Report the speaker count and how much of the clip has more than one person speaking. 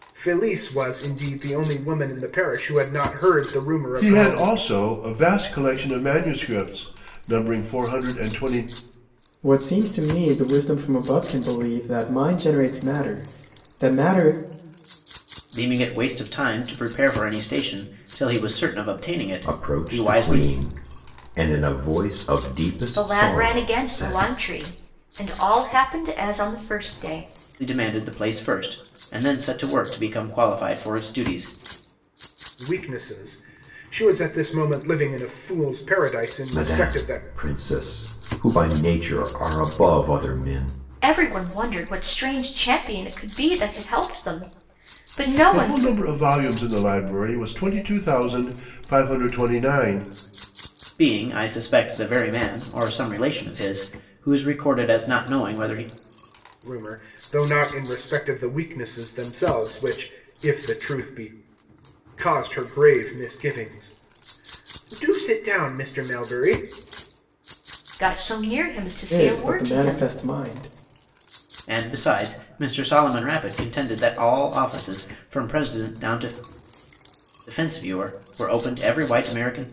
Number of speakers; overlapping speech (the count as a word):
six, about 7%